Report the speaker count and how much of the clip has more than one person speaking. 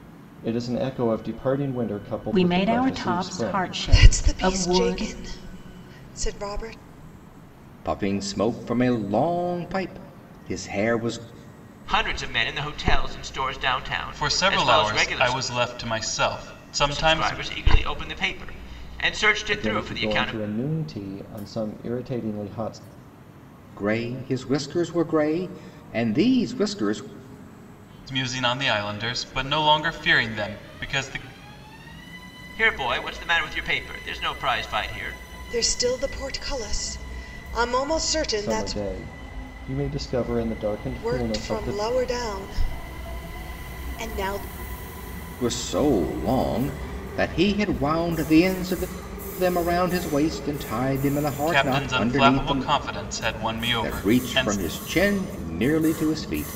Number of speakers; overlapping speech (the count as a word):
six, about 16%